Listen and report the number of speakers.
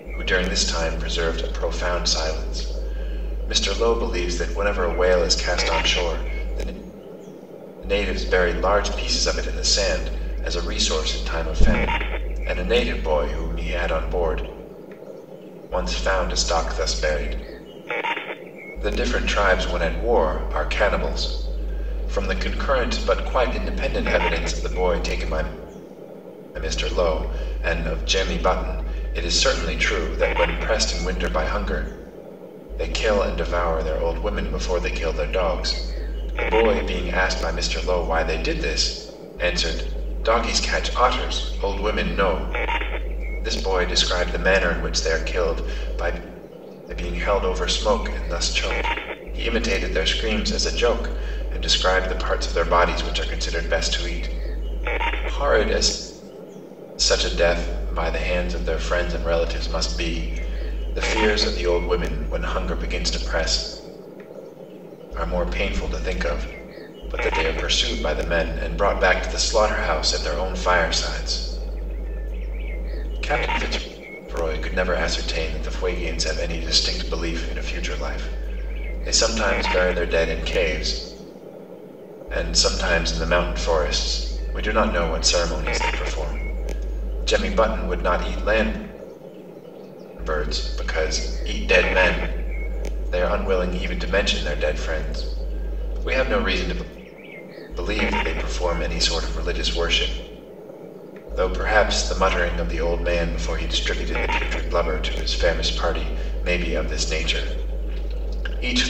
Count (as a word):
one